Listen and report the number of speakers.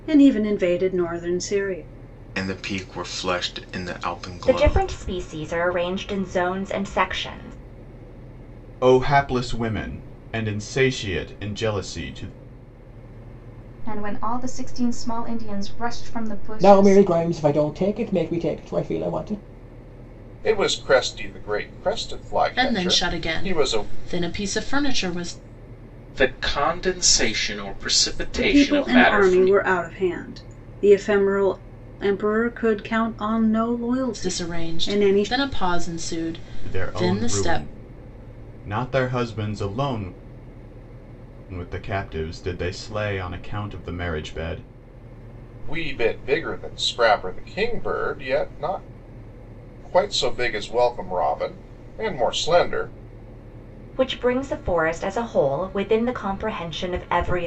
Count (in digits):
9